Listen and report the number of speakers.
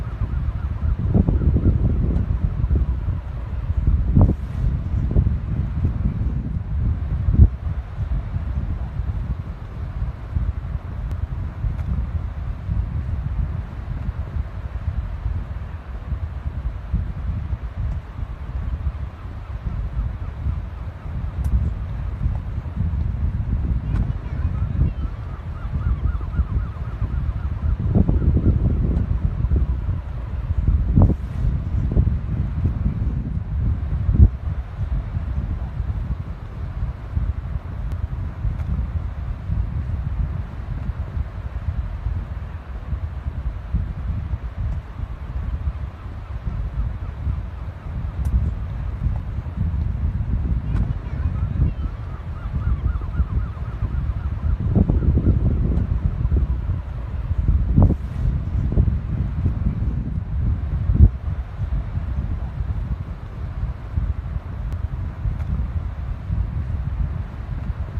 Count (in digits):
0